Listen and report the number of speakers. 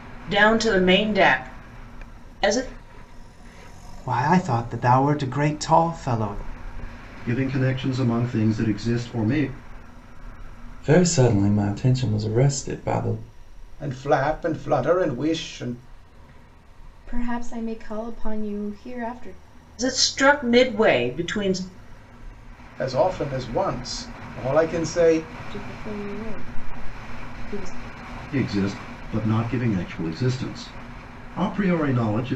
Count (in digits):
6